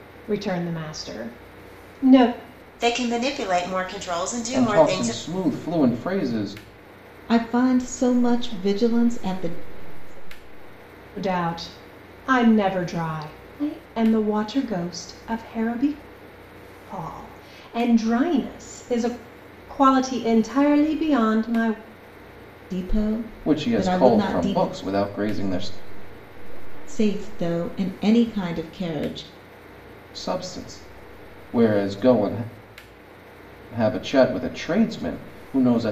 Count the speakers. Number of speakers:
five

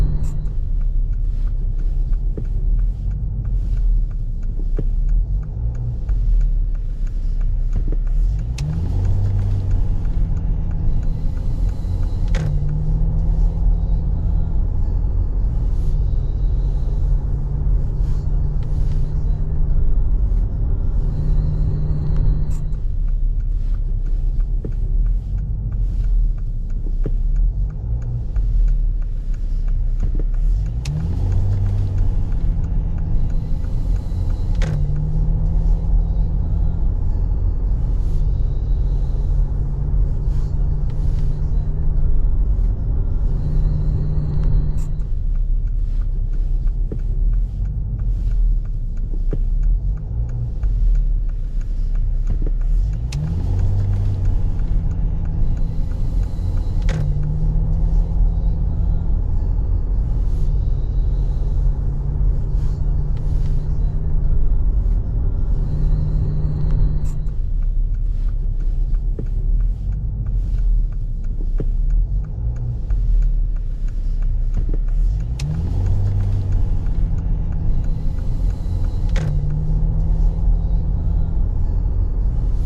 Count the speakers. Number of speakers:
zero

